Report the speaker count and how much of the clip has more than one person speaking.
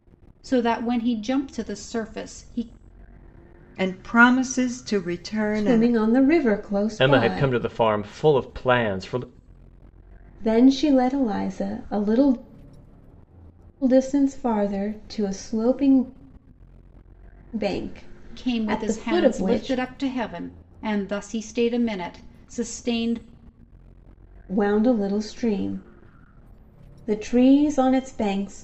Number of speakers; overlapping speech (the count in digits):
4, about 9%